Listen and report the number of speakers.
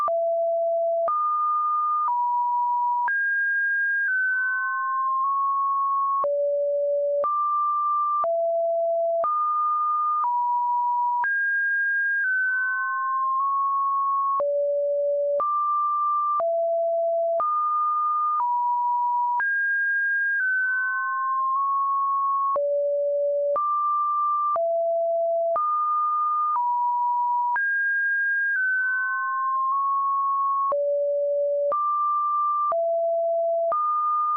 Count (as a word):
zero